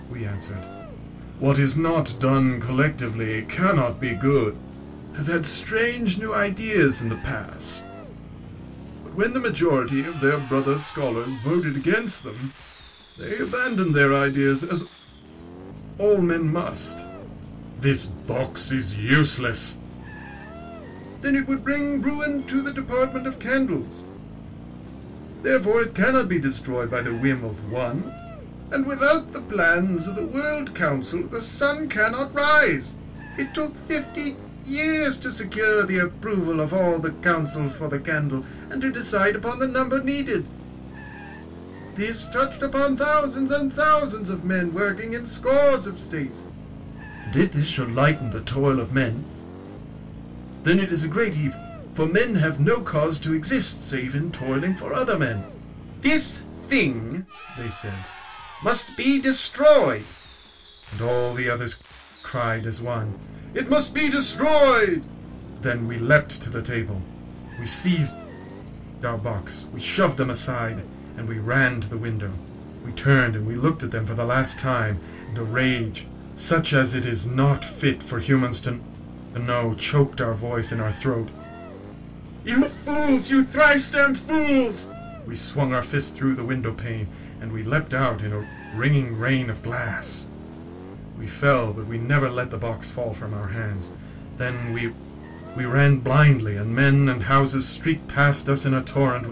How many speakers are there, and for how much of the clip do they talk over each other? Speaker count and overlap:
one, no overlap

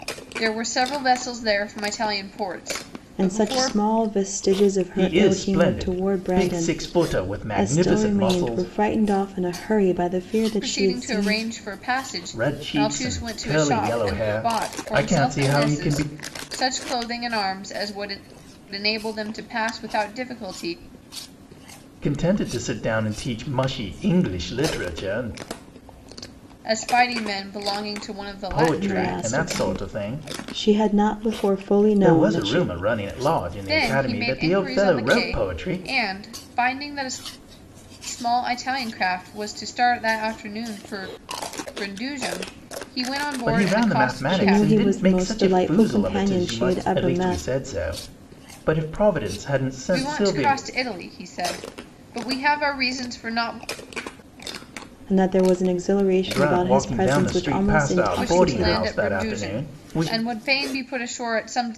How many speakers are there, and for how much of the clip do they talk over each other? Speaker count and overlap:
three, about 35%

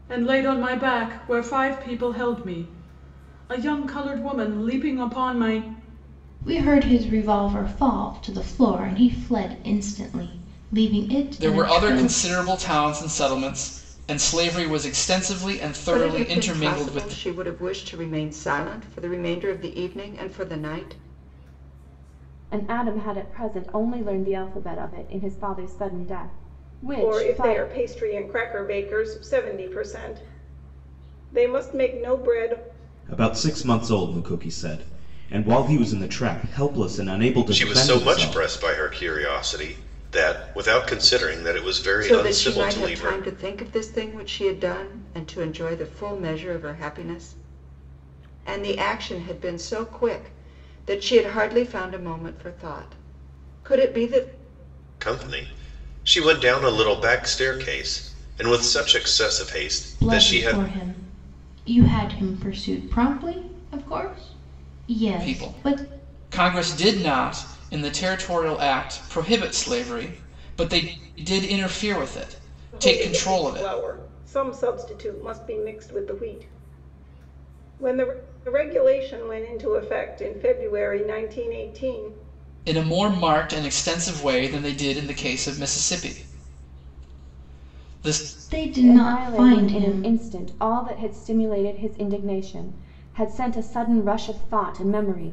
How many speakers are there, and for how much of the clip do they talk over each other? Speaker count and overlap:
eight, about 9%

